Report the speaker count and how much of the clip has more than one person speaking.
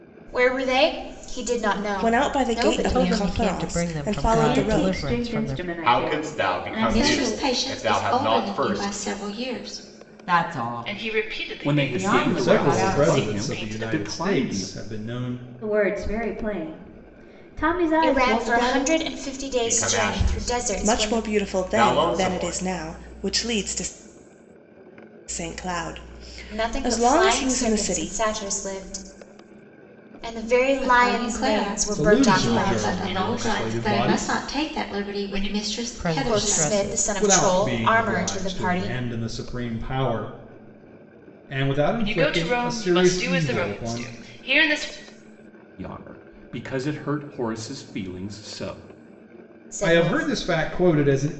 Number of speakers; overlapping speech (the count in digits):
10, about 52%